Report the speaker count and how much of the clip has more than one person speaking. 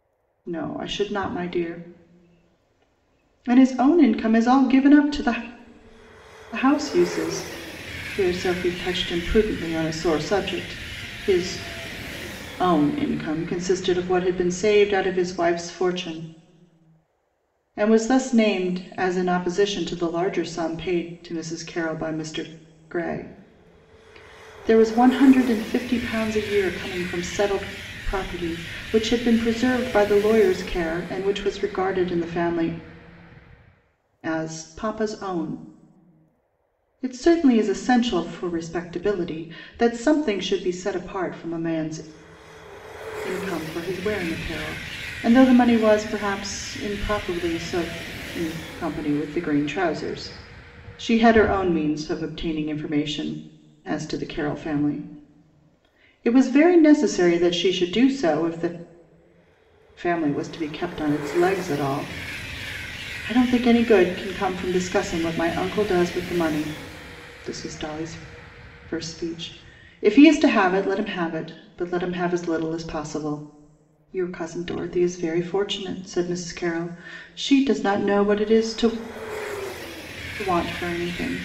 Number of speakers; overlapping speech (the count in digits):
1, no overlap